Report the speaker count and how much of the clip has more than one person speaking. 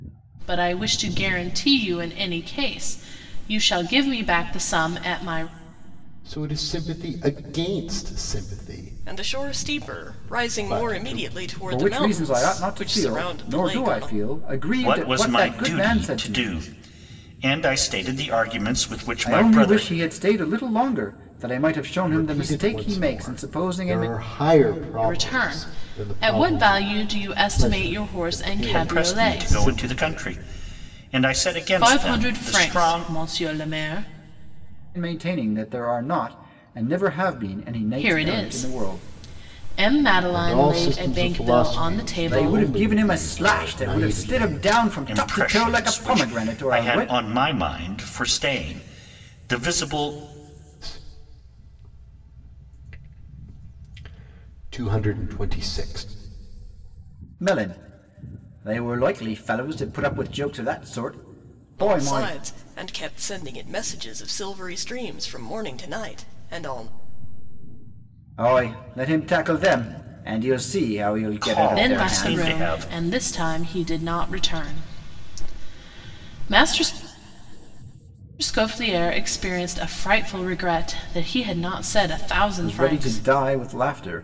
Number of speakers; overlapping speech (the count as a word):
five, about 31%